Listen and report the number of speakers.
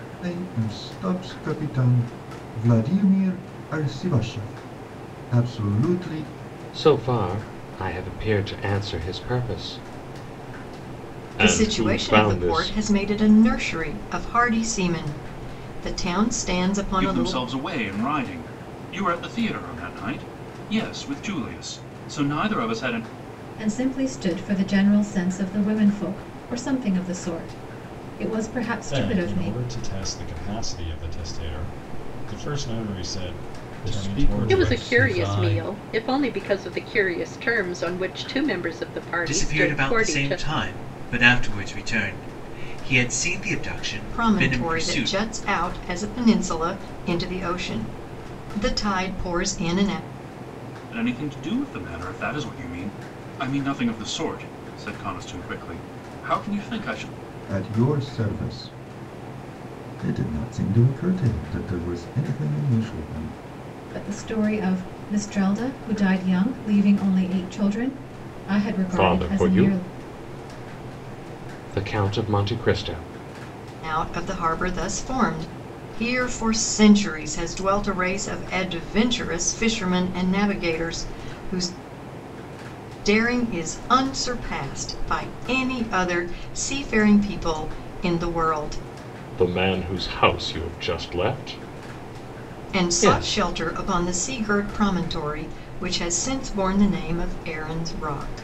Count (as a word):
nine